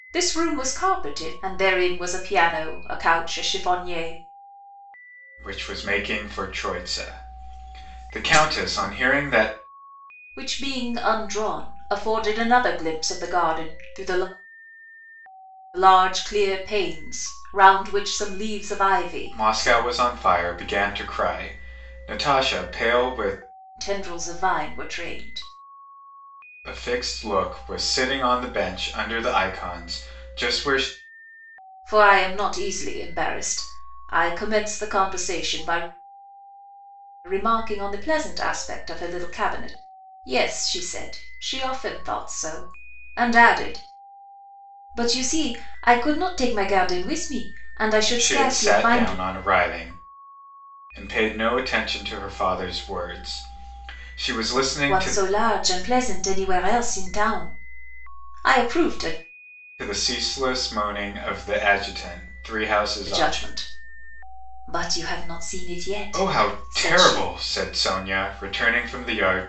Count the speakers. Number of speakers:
two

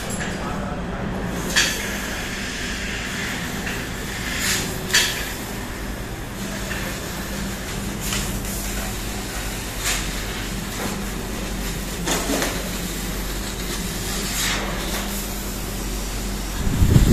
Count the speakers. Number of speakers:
zero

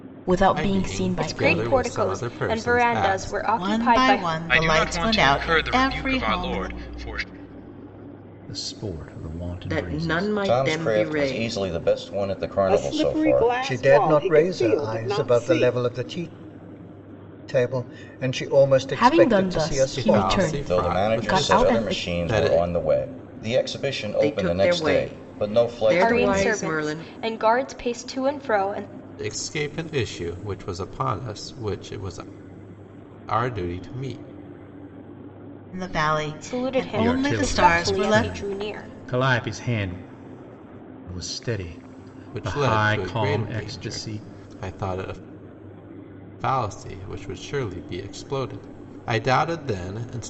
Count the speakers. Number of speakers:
ten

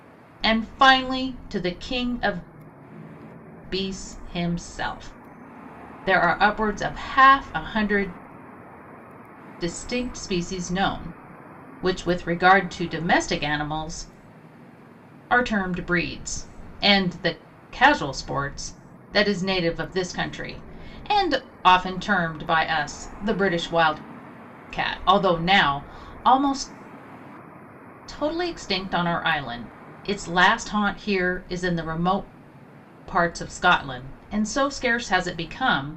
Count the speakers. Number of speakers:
one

